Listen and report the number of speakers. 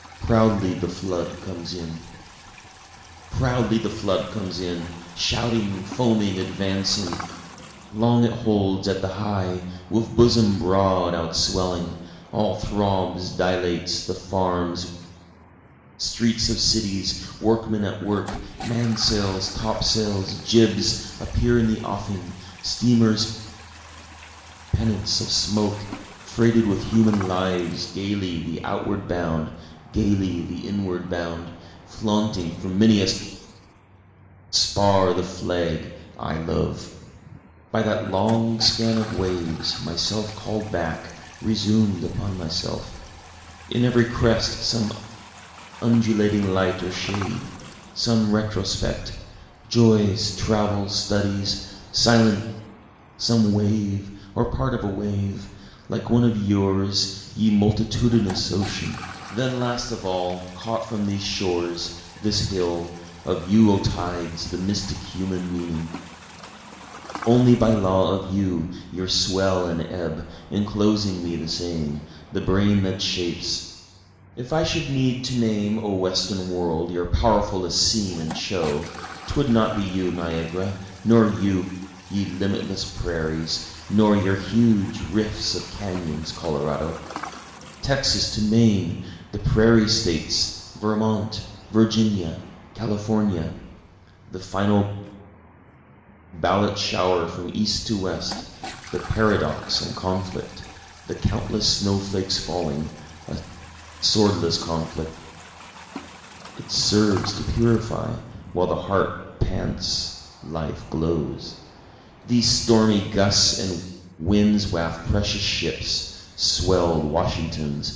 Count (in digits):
1